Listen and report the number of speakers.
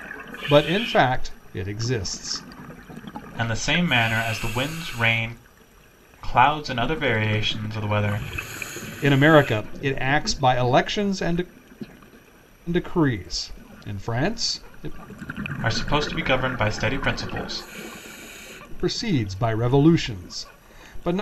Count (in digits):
2